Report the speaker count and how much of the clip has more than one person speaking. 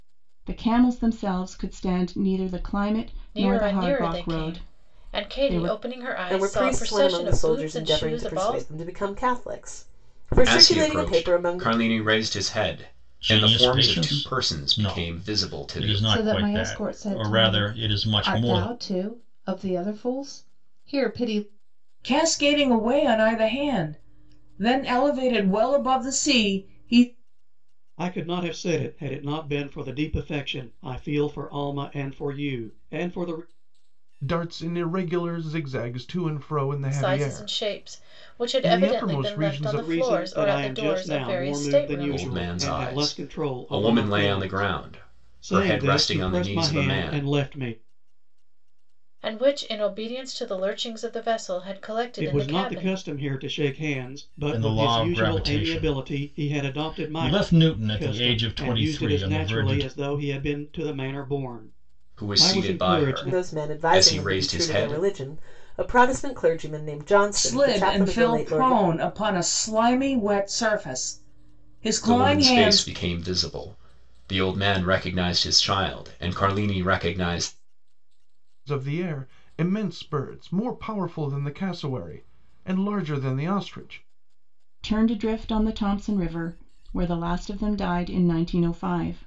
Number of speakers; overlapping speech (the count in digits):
9, about 36%